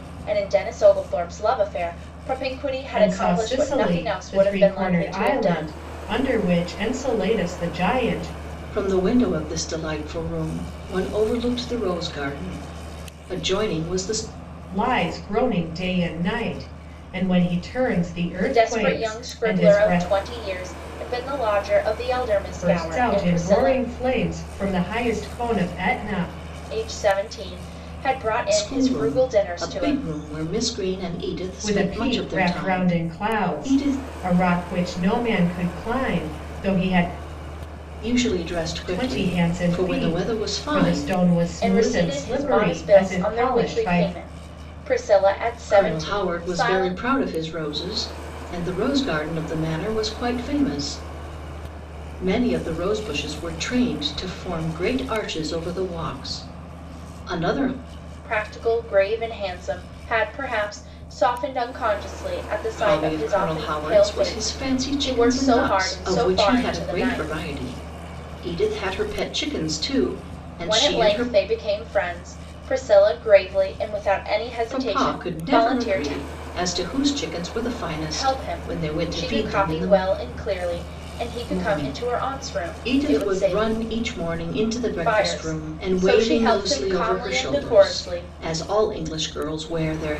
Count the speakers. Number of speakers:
3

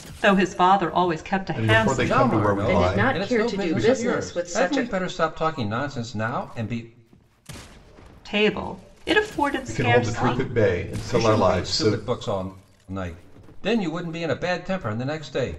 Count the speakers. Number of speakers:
4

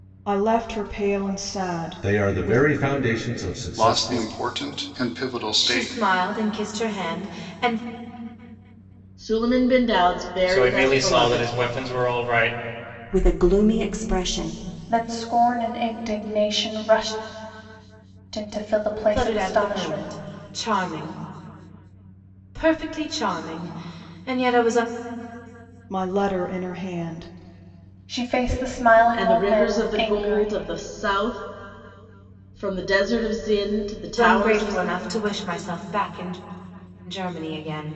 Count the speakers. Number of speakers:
8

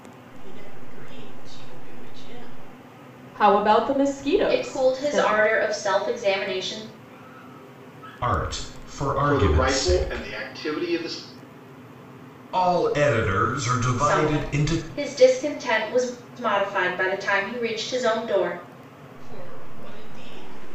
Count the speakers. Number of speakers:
5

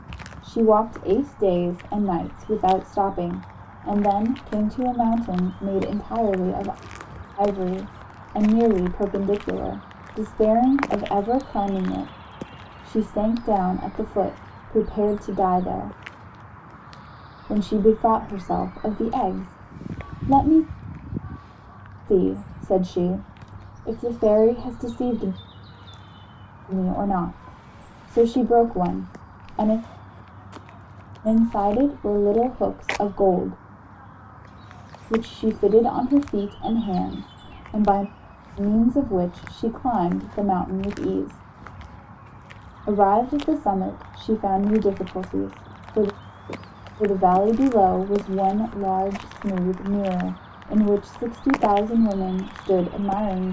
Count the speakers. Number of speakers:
1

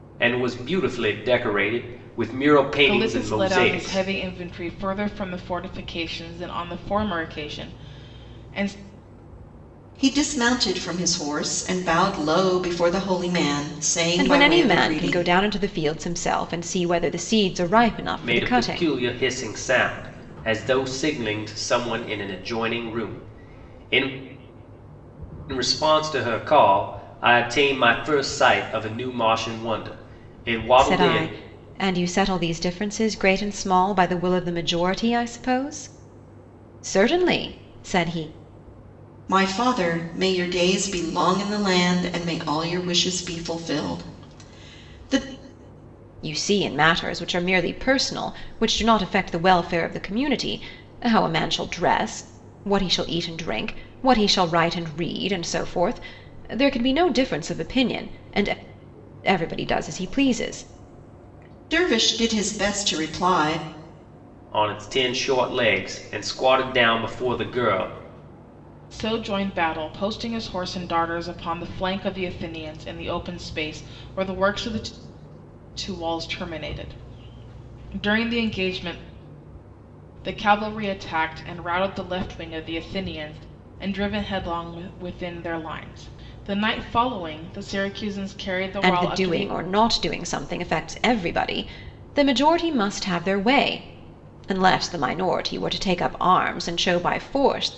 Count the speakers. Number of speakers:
4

